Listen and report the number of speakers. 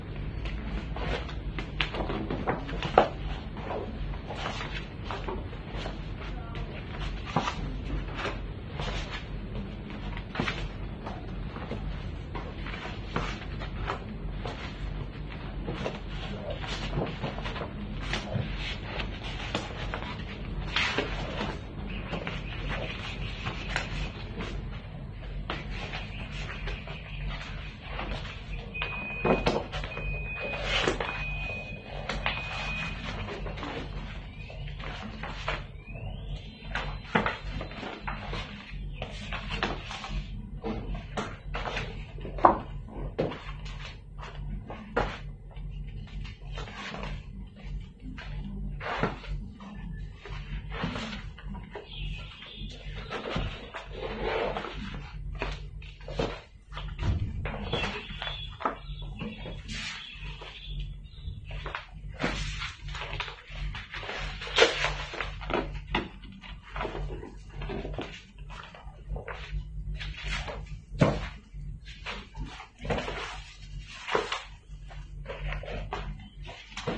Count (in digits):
0